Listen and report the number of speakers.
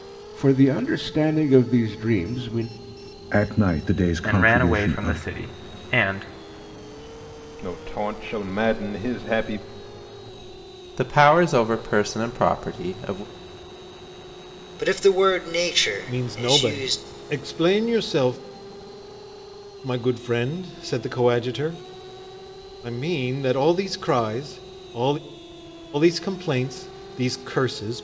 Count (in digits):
7